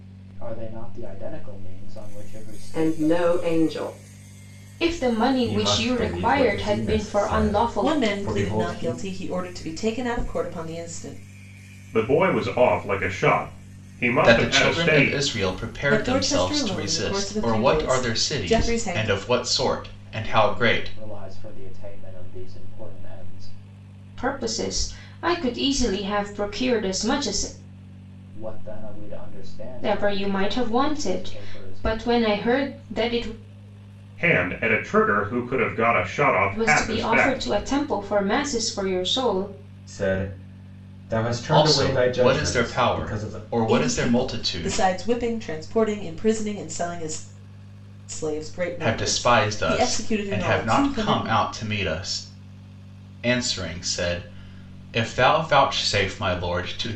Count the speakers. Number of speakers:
7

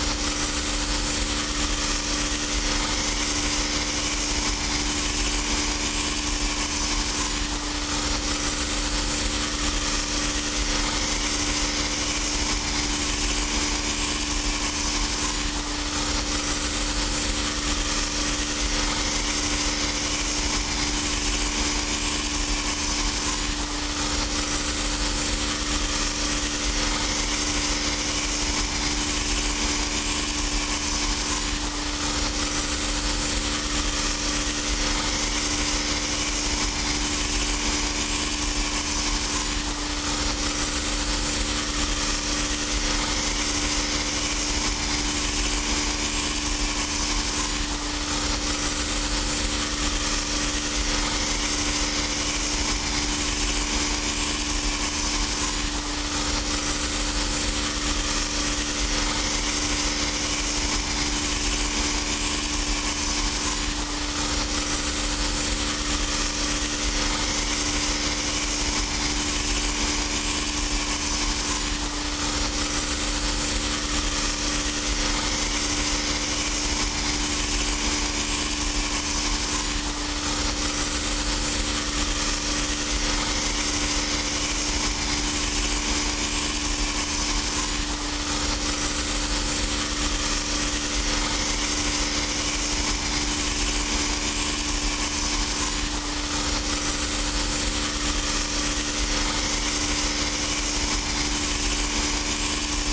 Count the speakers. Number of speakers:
0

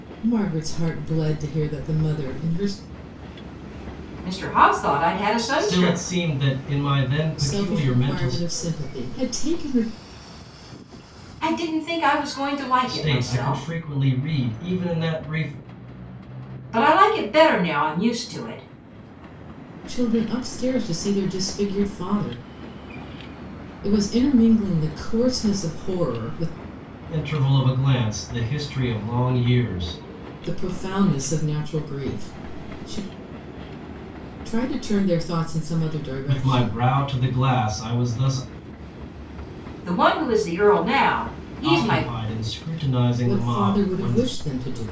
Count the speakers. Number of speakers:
3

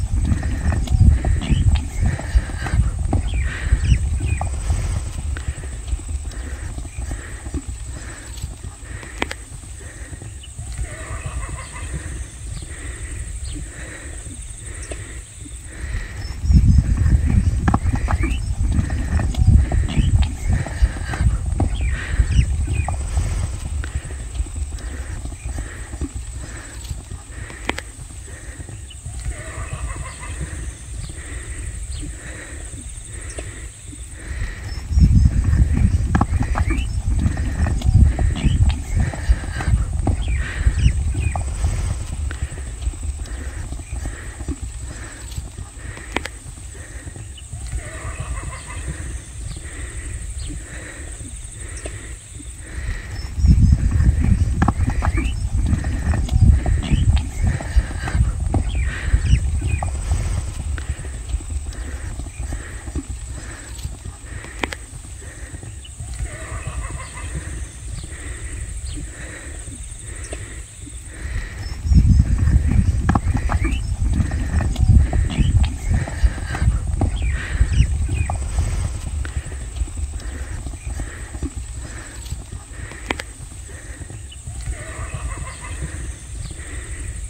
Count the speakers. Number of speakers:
0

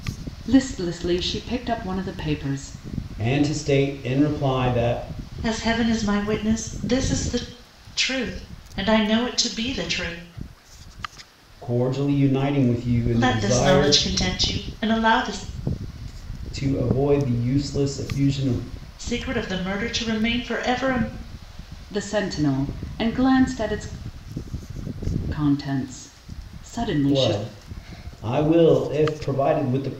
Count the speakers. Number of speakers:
3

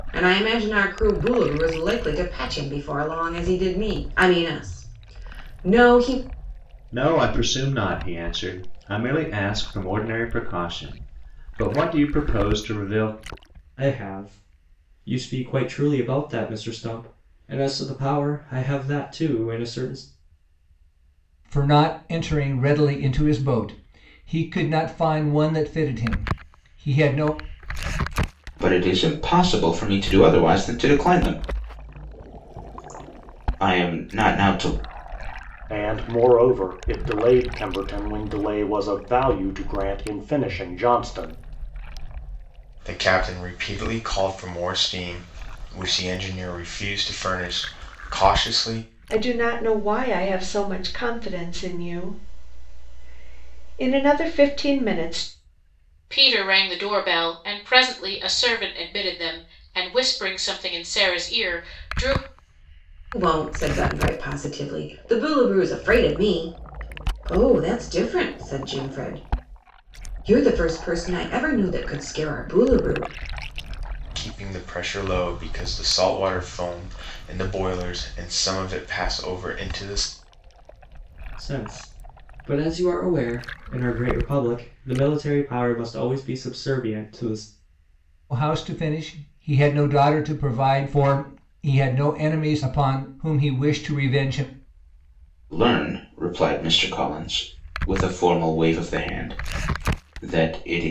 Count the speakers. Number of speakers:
9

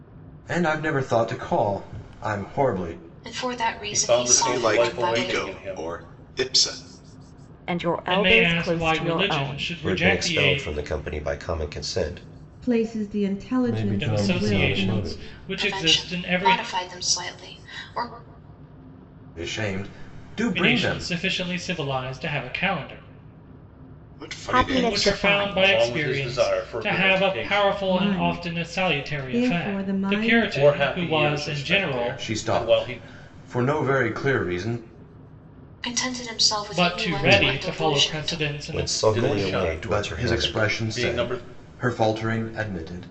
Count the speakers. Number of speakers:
9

